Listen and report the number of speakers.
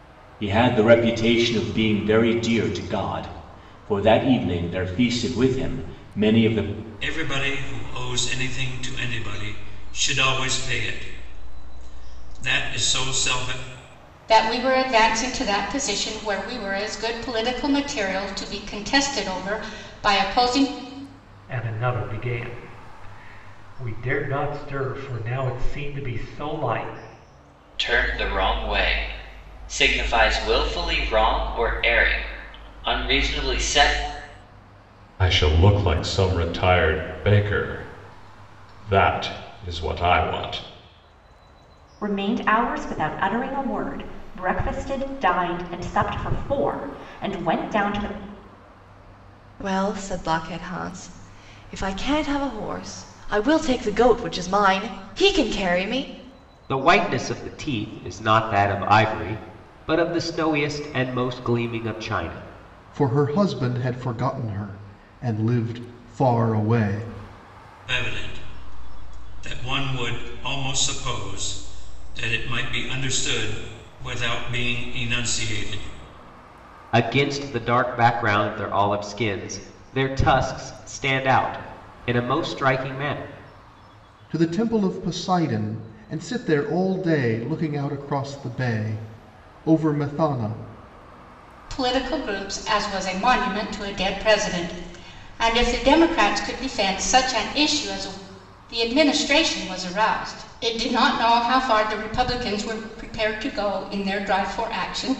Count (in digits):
10